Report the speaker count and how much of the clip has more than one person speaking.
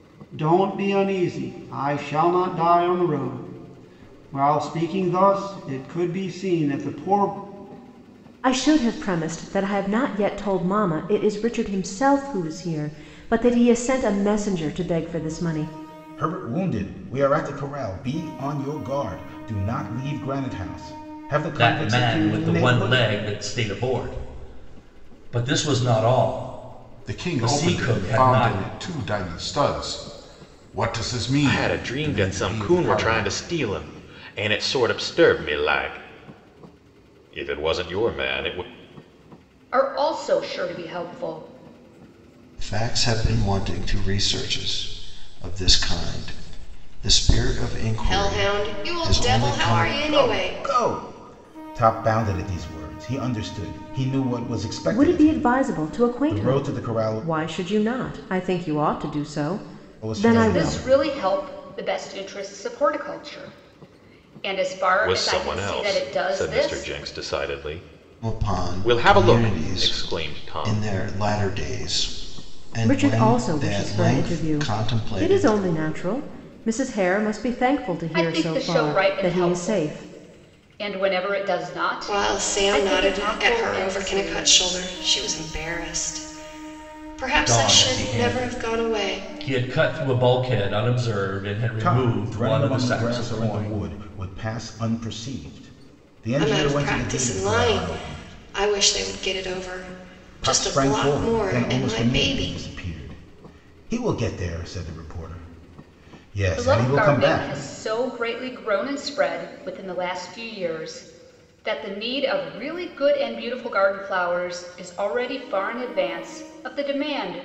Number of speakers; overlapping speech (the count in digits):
9, about 27%